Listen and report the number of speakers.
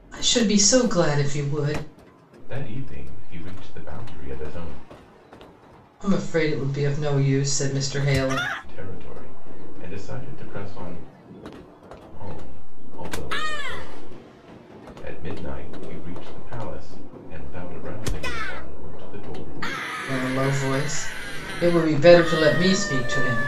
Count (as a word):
two